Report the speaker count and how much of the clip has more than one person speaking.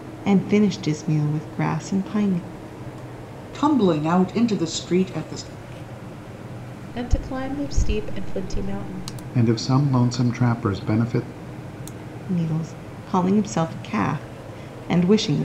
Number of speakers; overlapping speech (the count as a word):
four, no overlap